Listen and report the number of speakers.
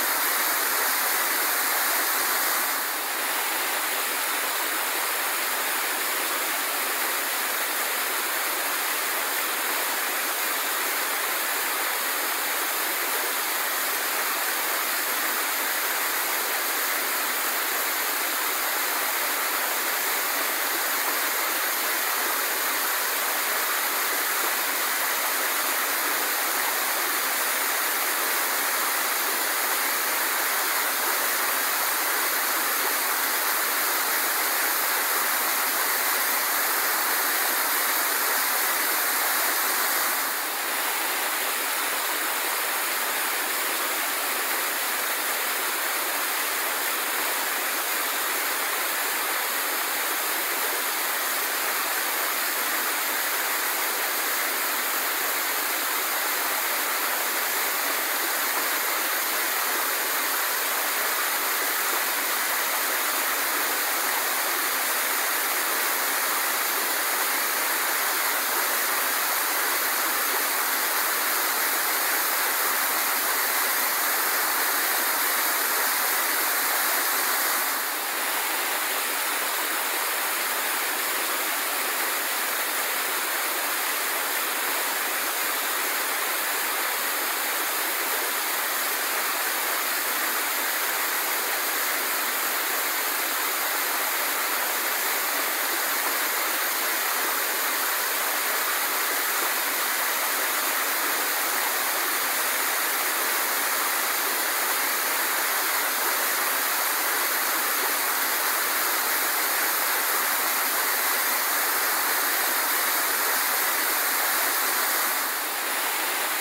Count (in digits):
0